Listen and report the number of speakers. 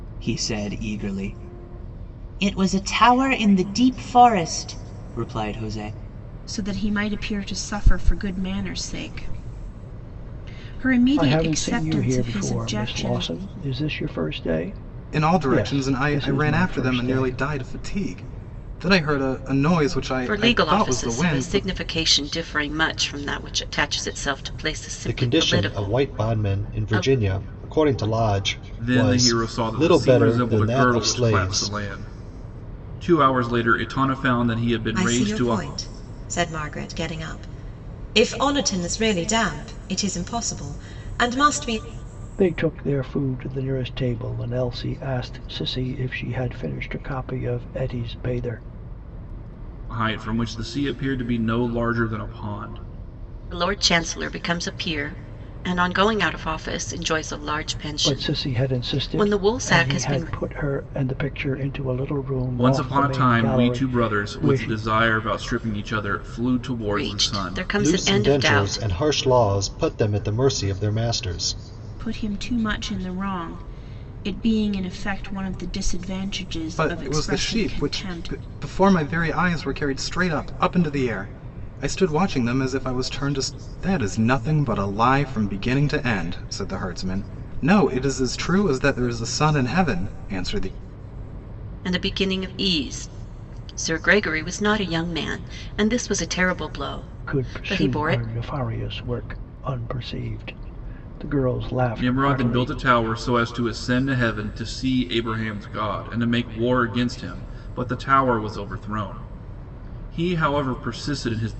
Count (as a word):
eight